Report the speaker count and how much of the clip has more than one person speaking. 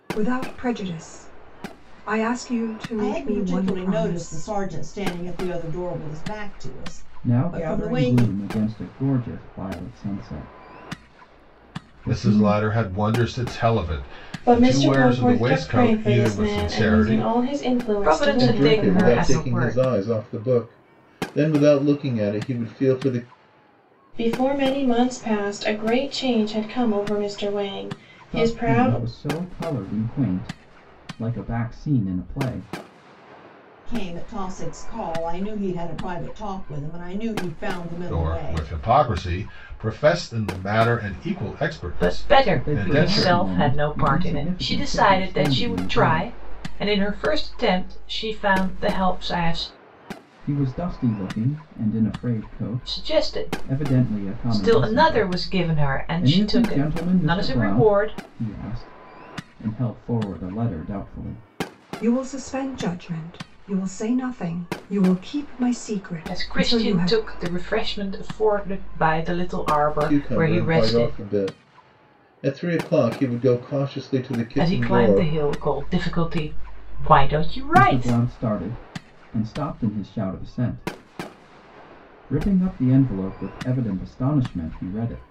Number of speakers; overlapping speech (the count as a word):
seven, about 25%